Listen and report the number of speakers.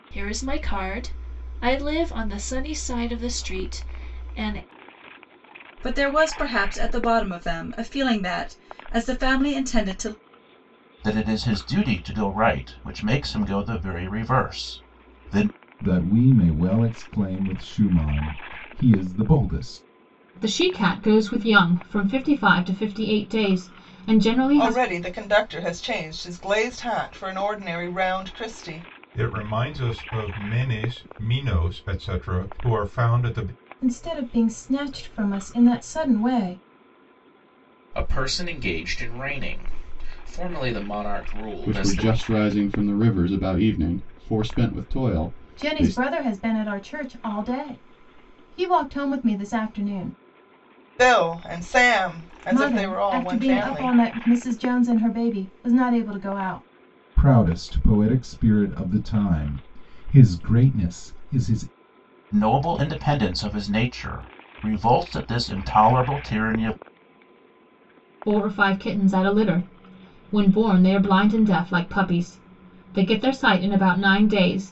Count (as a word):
ten